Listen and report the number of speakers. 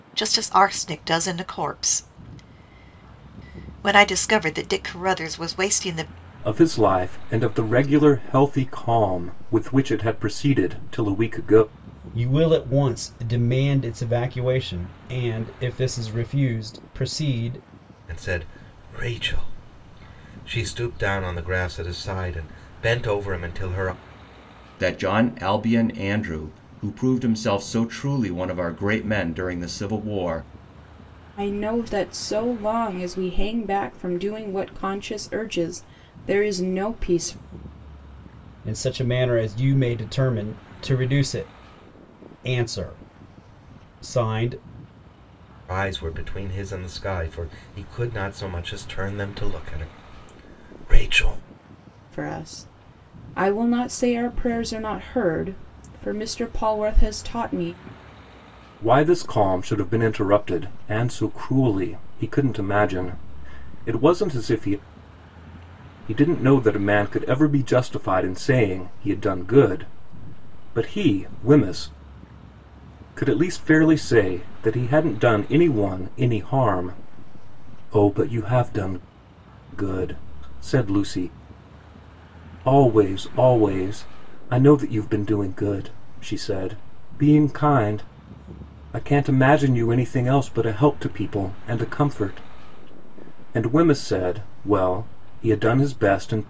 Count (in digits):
6